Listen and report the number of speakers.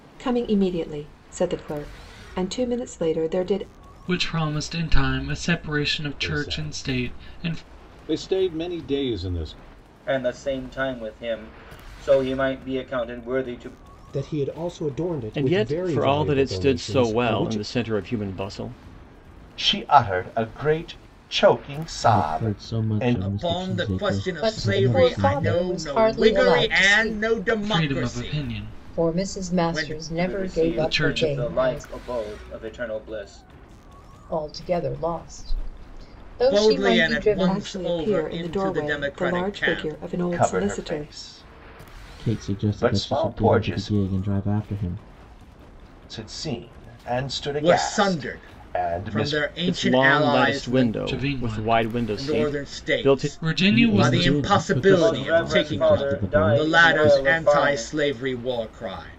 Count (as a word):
ten